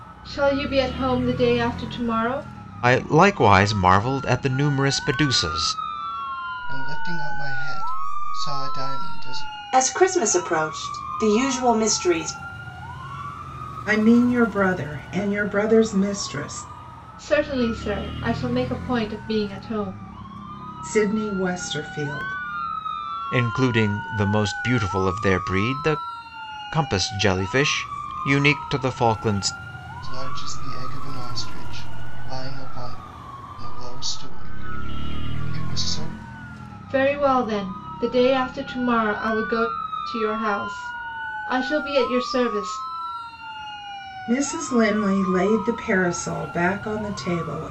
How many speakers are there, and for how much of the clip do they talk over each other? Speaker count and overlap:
5, no overlap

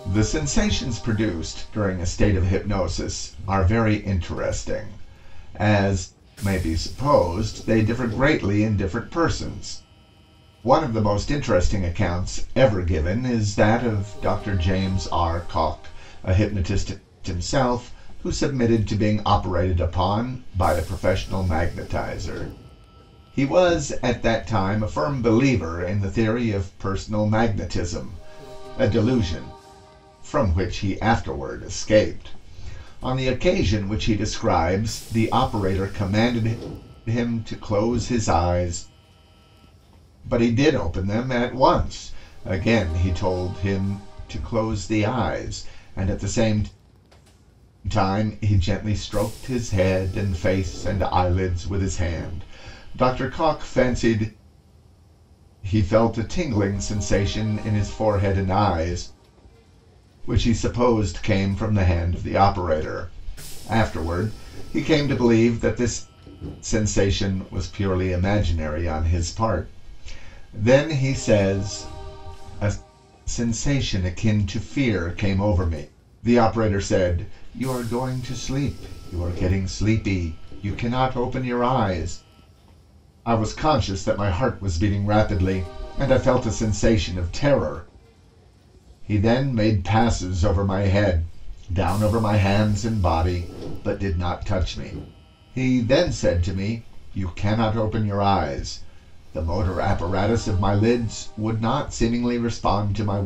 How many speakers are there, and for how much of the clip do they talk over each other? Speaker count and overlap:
1, no overlap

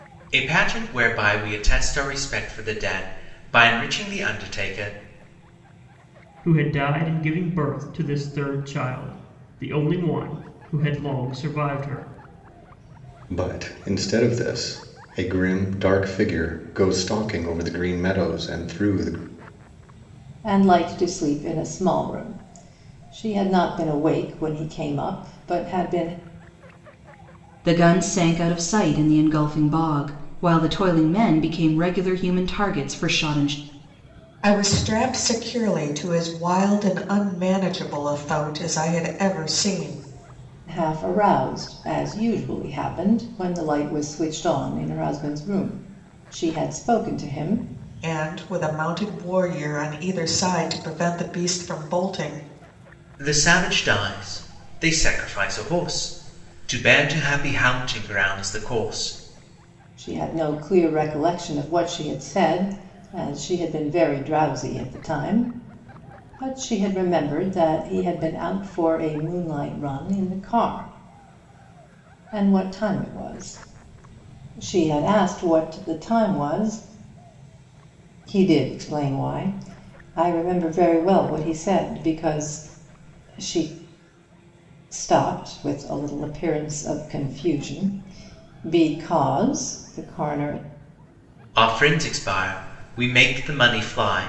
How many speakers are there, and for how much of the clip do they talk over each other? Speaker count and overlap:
6, no overlap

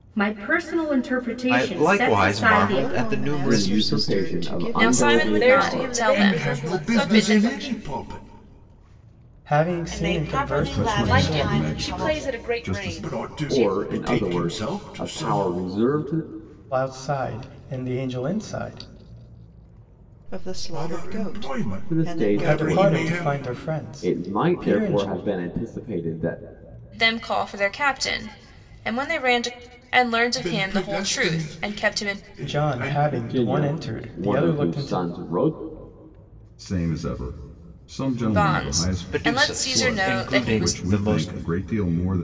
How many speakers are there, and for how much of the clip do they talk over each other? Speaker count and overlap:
10, about 57%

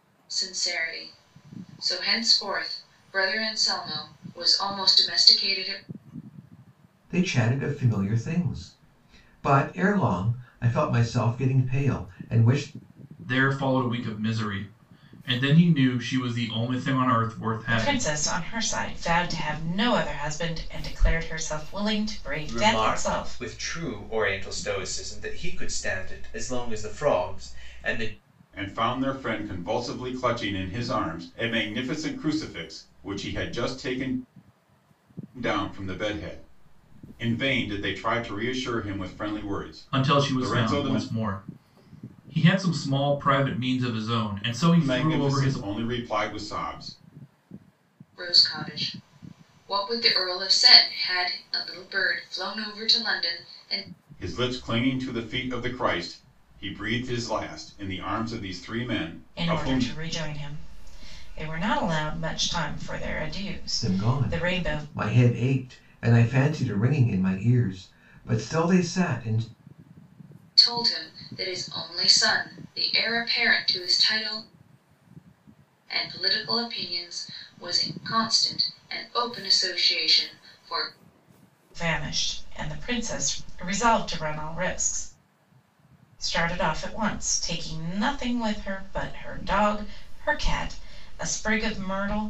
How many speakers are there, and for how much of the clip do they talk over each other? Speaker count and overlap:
6, about 5%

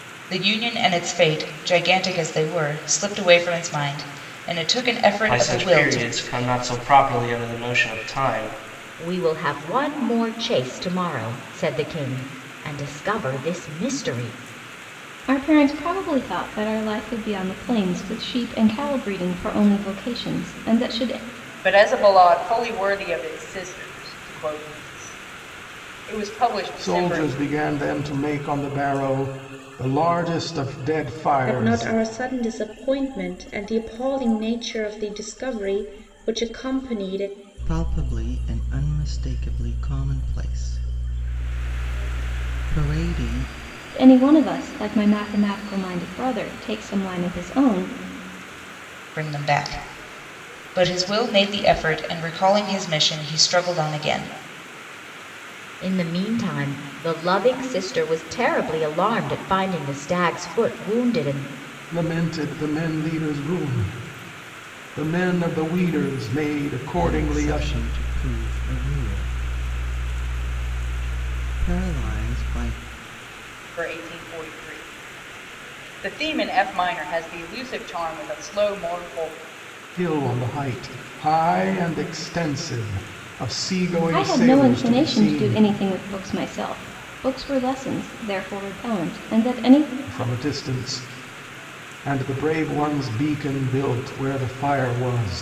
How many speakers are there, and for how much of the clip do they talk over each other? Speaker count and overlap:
8, about 4%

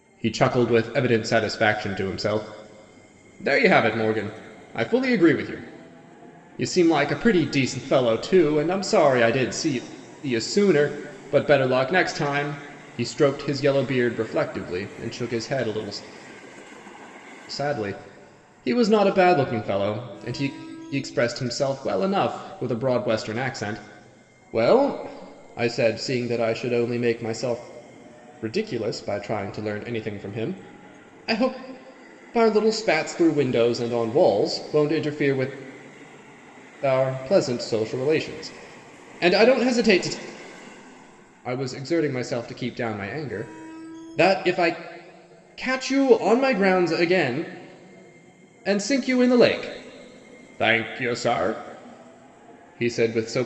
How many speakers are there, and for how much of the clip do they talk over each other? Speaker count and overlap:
1, no overlap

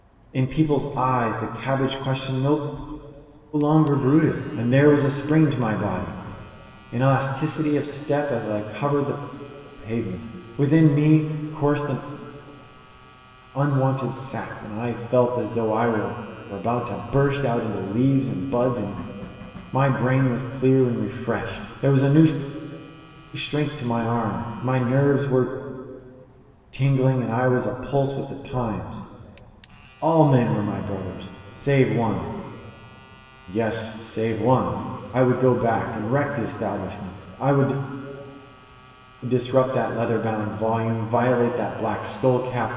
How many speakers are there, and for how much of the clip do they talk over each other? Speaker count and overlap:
1, no overlap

